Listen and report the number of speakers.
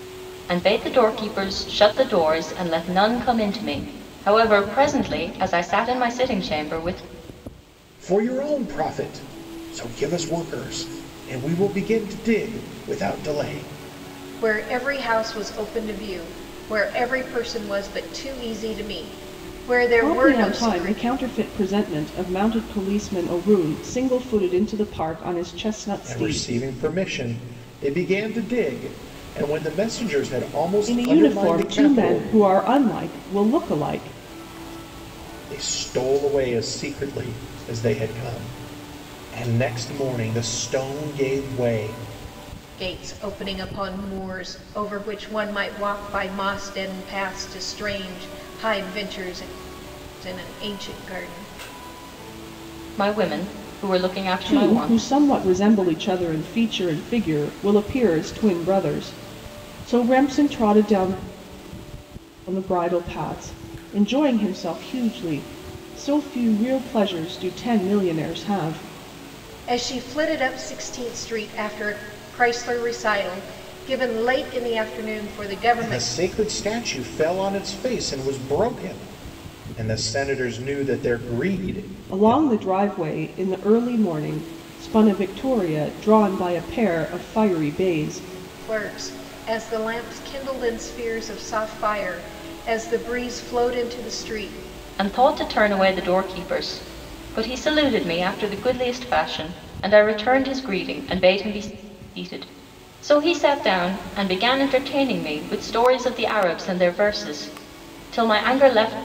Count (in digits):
4